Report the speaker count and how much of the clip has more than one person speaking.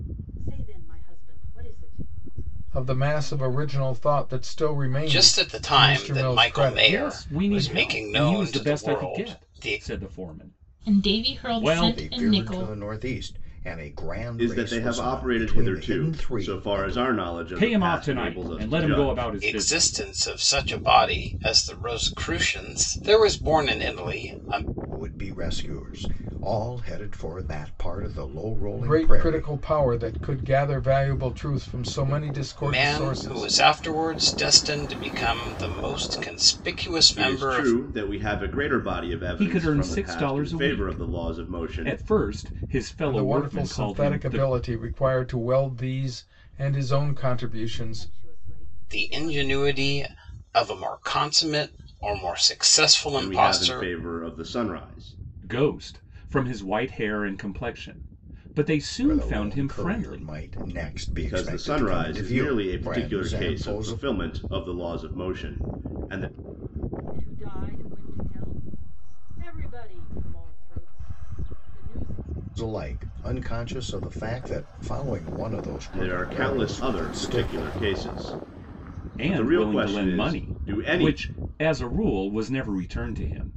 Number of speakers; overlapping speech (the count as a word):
seven, about 38%